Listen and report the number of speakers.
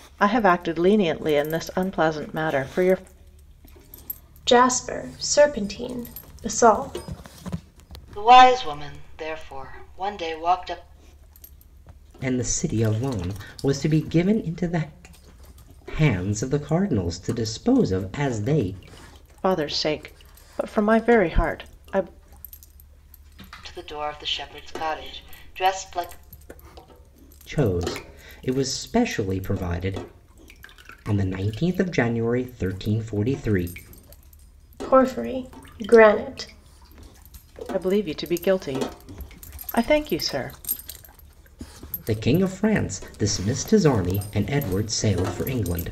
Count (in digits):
4